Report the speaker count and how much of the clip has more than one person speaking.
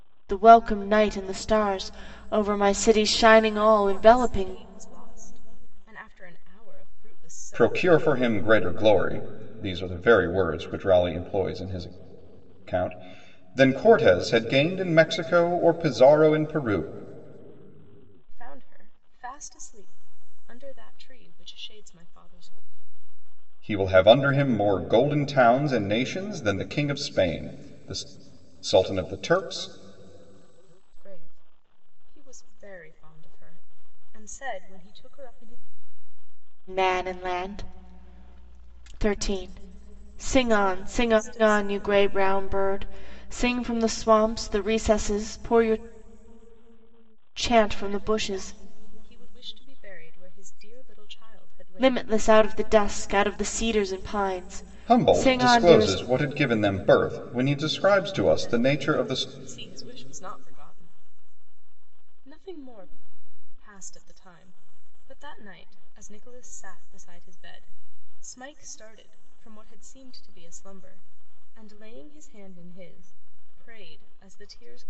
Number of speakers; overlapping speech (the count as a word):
three, about 9%